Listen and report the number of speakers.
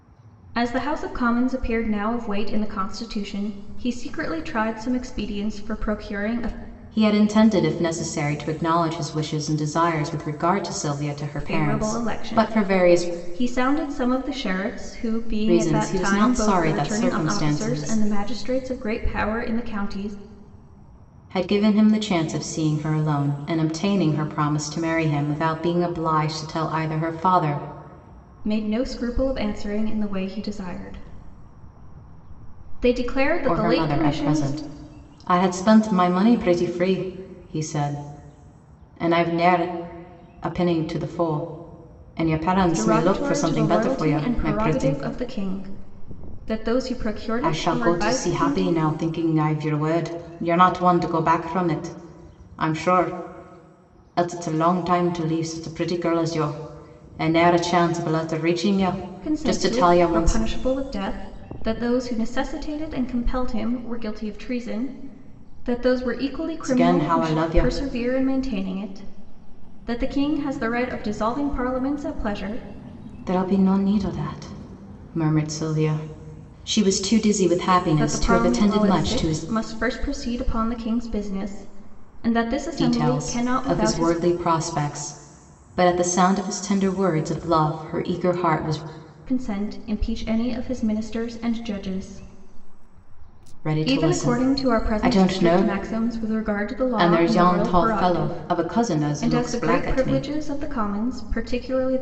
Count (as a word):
two